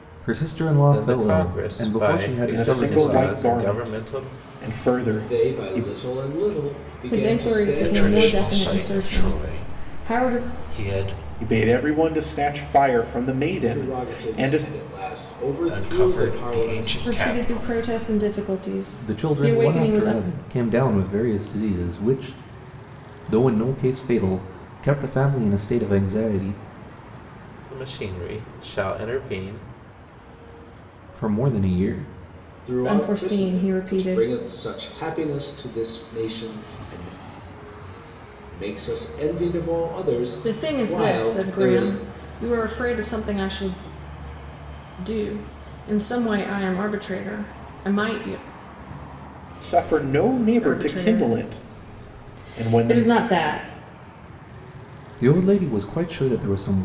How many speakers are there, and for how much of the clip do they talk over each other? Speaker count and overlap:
six, about 30%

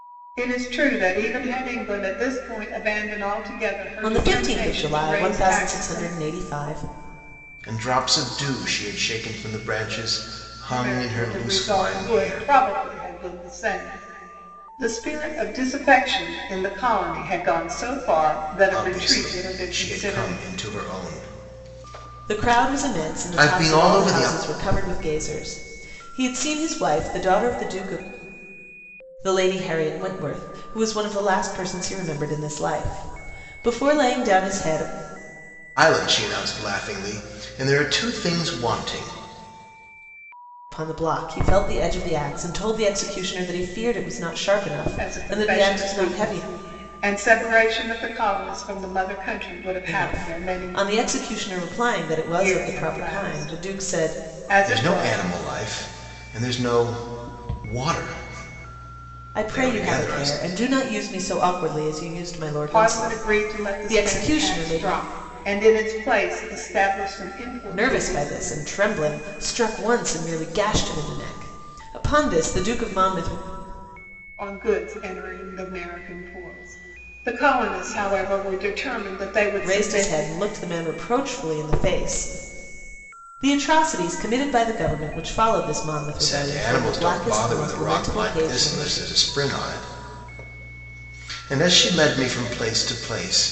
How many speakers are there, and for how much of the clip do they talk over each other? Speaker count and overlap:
three, about 21%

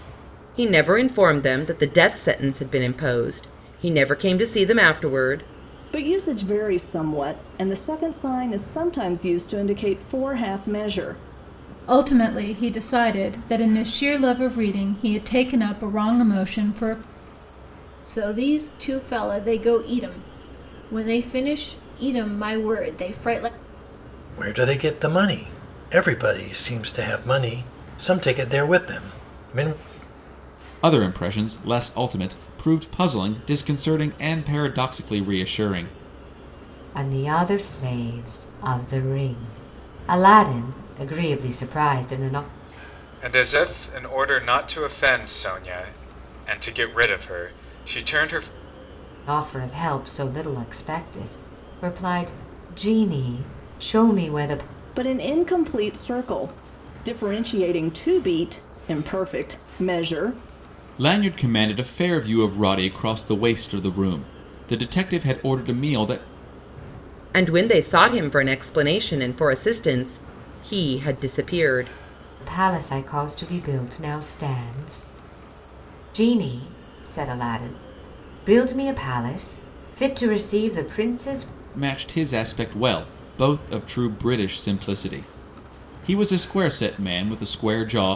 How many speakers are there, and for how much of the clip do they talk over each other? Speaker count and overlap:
eight, no overlap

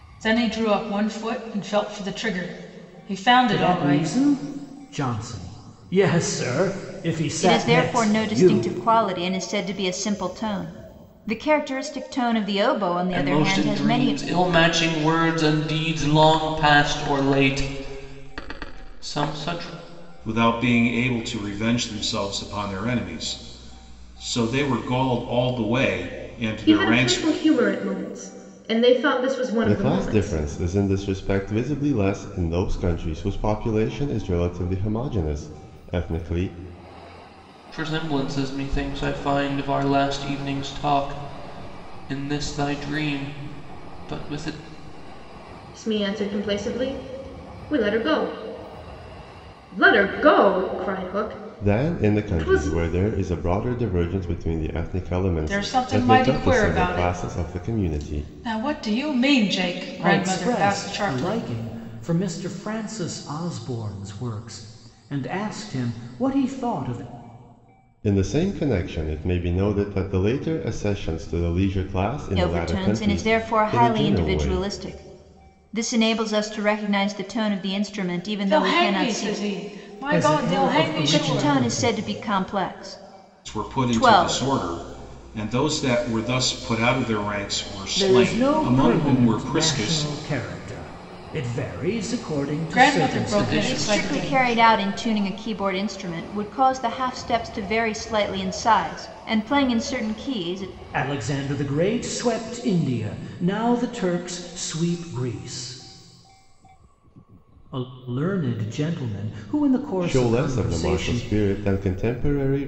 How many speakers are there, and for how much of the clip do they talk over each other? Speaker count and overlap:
seven, about 19%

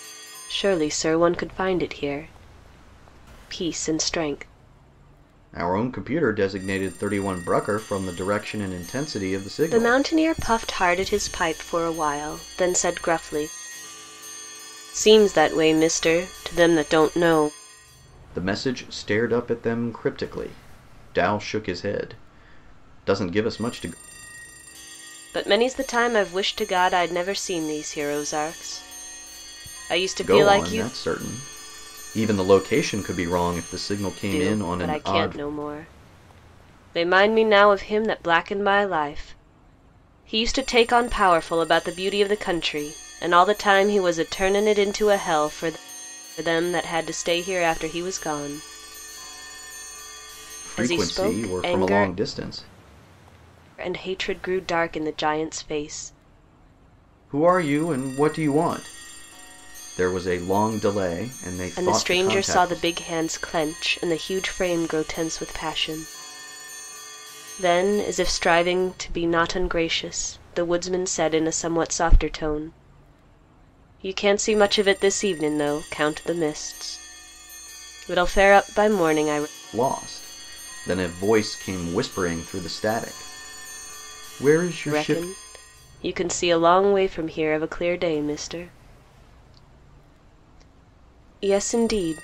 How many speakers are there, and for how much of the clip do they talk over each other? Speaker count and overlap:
two, about 6%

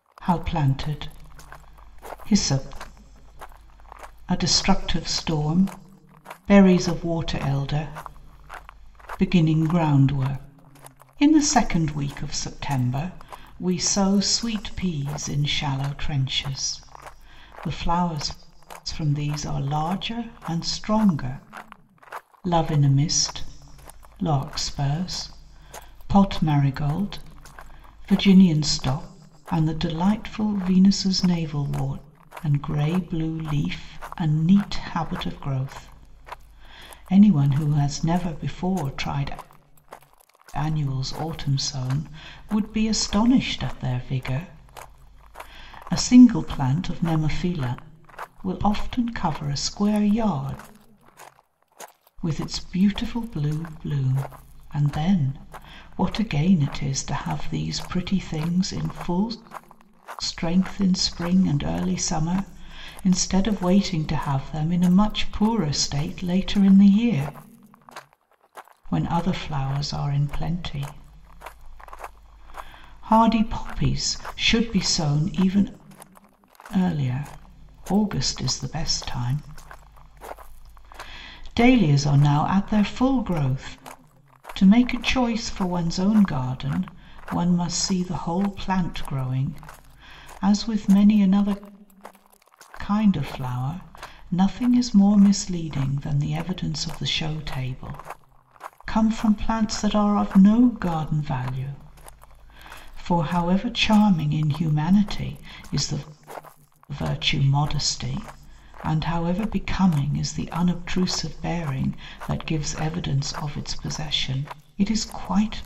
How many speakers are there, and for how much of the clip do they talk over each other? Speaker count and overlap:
one, no overlap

